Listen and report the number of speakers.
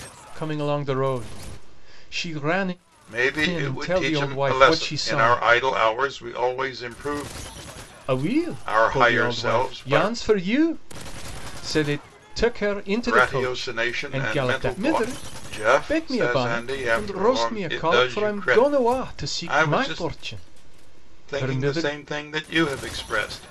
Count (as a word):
two